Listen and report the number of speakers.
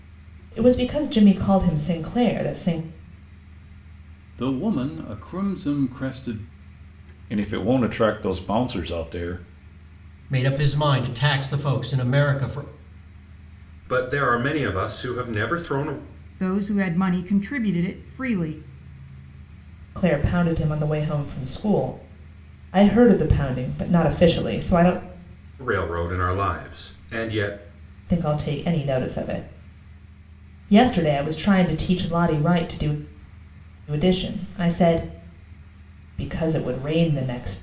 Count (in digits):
6